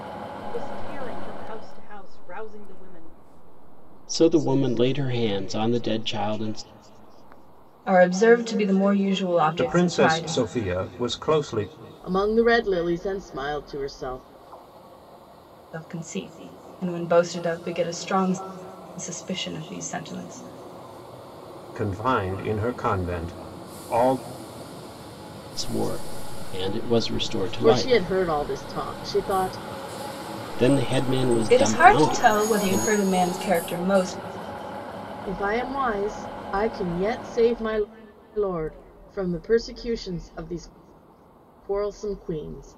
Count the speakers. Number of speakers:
five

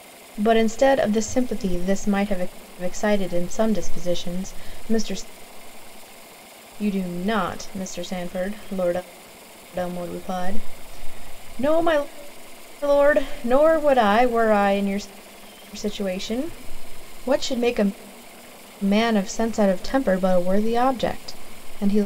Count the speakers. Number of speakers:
one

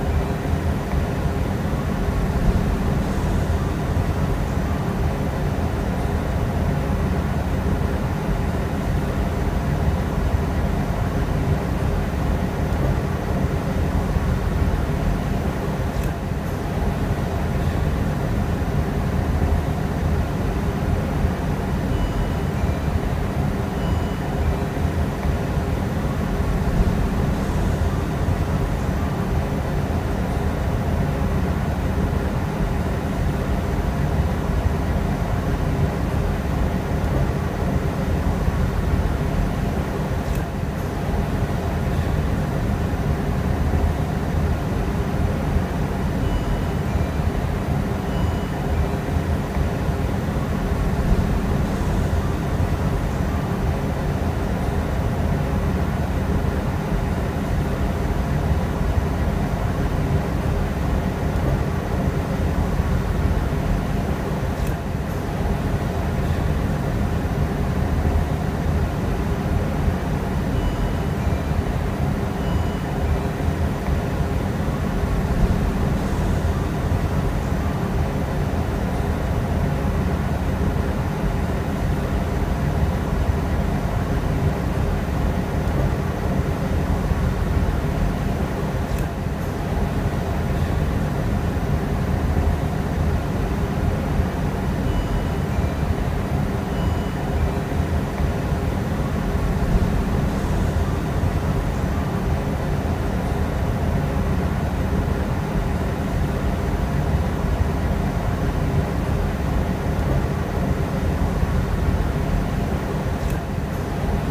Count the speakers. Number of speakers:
zero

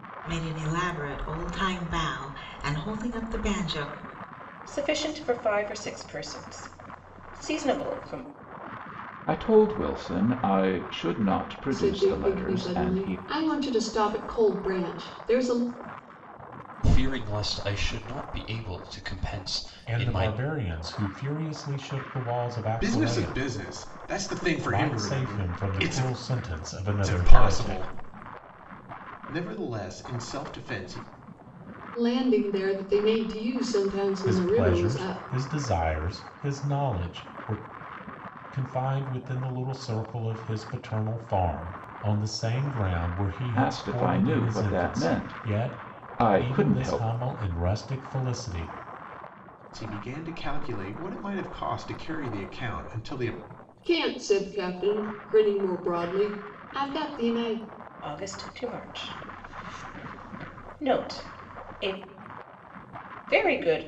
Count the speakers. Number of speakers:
seven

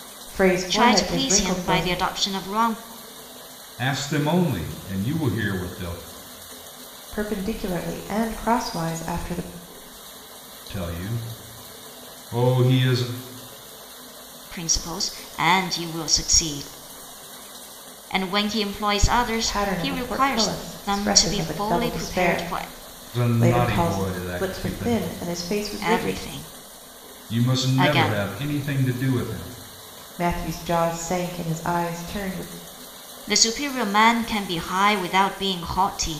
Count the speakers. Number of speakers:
three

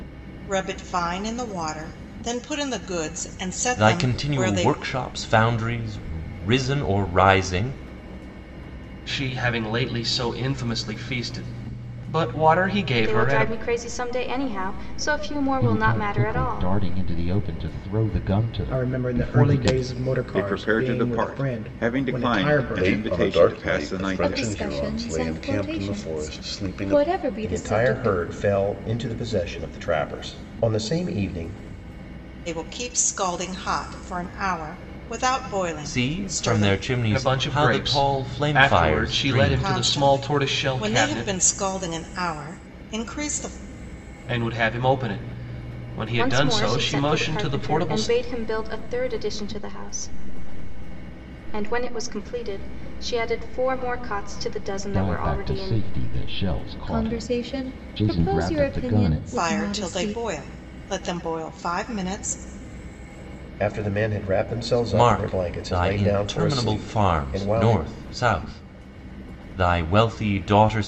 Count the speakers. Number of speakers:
ten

